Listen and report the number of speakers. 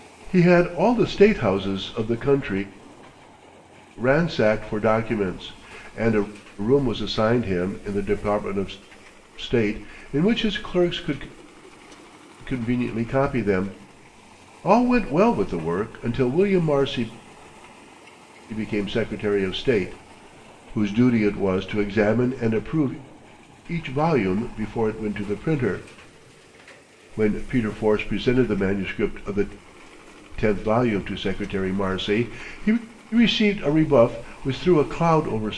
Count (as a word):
one